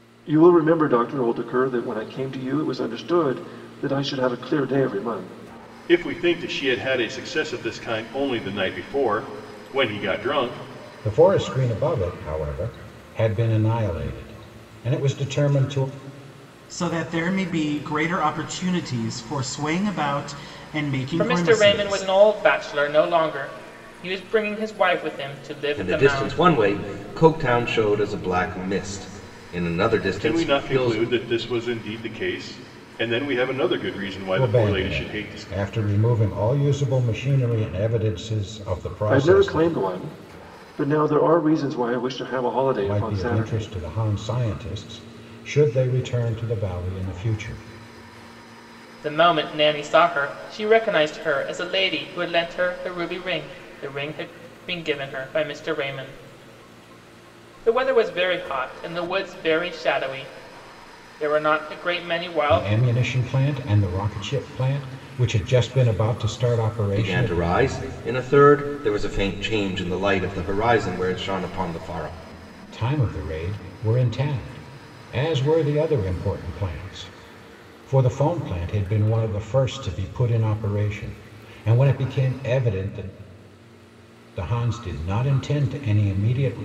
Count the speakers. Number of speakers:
6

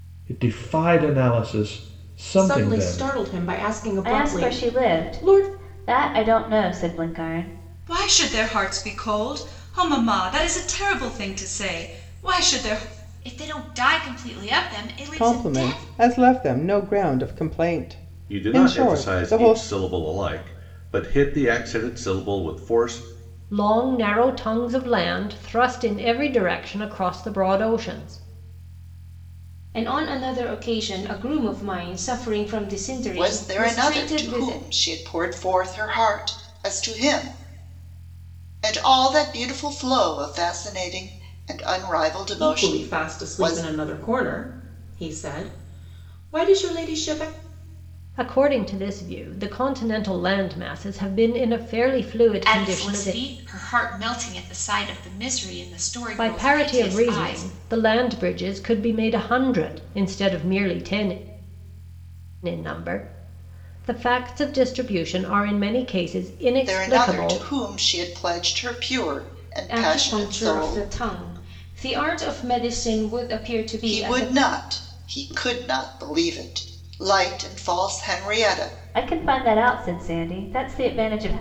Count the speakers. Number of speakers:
10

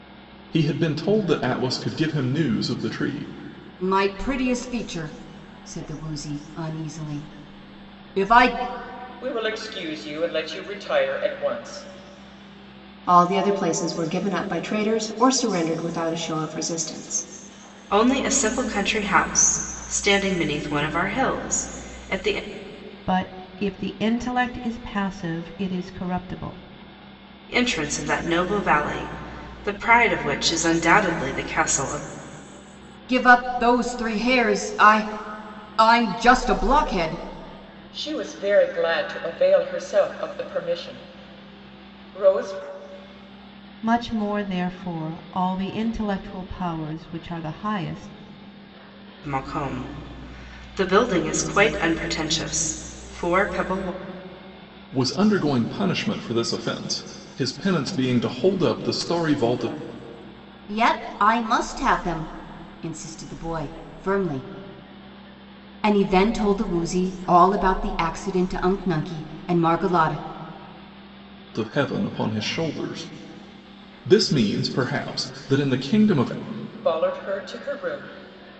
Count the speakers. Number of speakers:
6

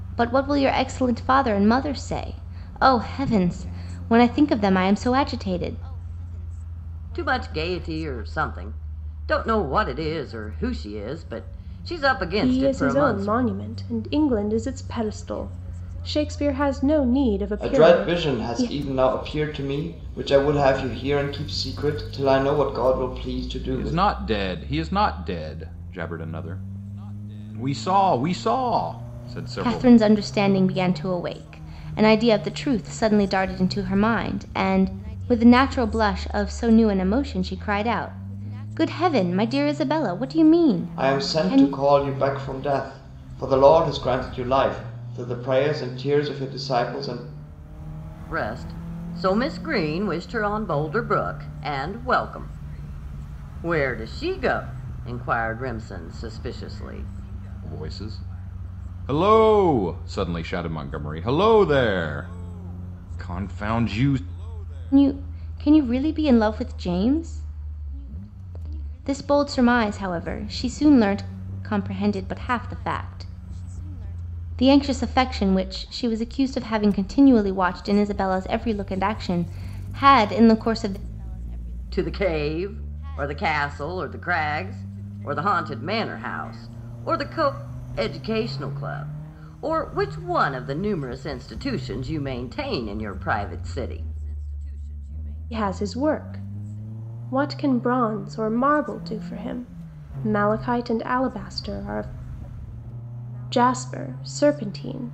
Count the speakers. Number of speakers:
5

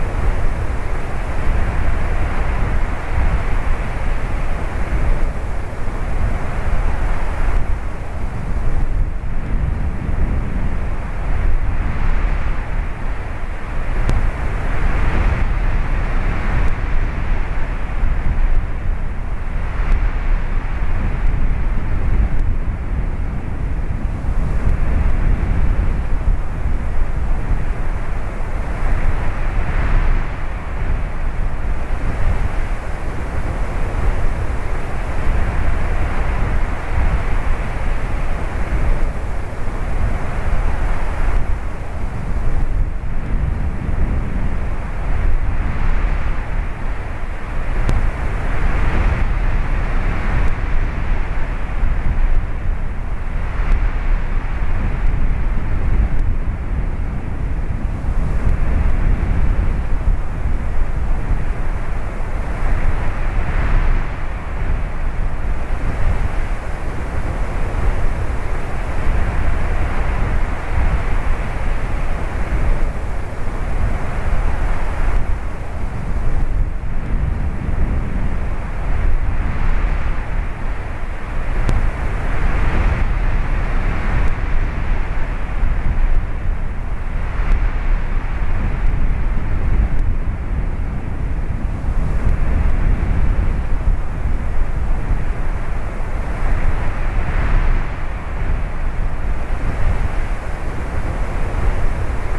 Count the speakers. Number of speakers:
0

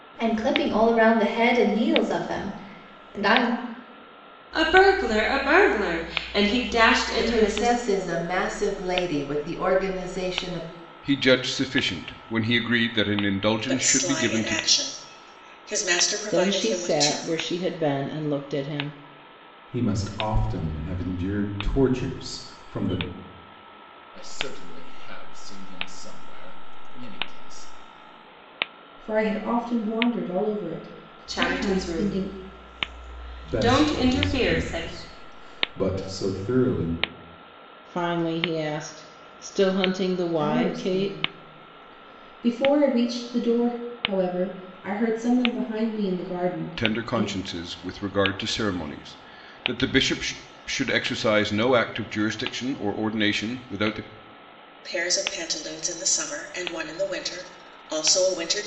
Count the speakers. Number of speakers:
9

